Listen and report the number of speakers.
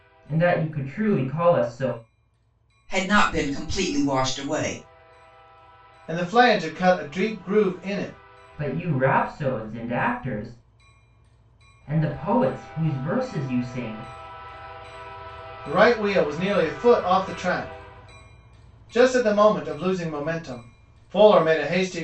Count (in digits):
3